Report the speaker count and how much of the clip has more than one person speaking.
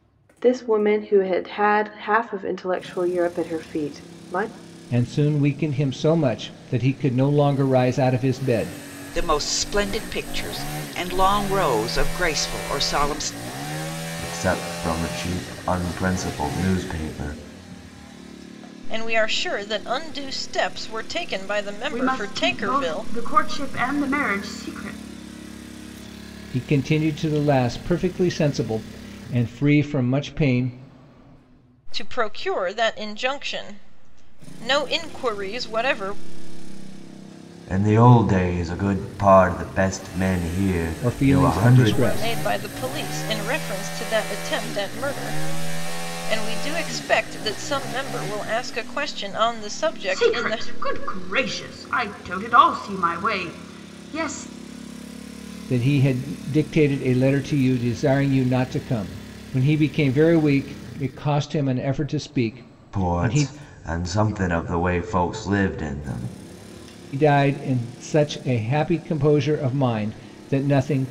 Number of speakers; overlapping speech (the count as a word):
six, about 5%